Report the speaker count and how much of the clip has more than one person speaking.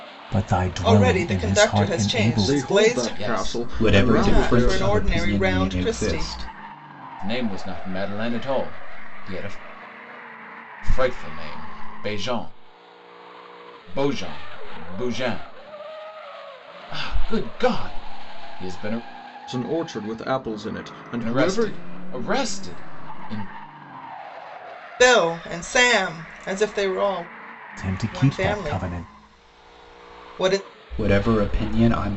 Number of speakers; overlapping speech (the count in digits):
5, about 22%